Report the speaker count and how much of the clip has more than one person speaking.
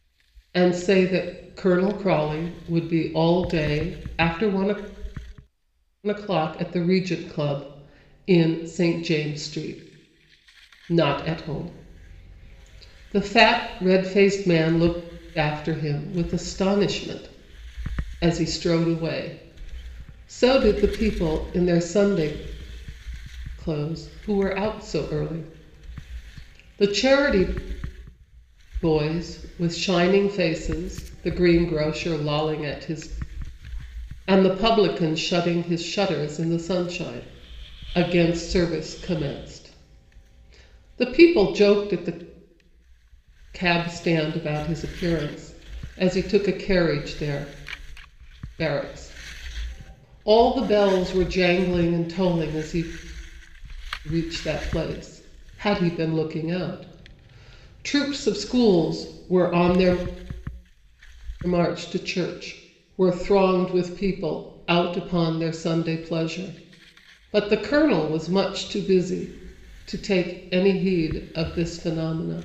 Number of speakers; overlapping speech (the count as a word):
one, no overlap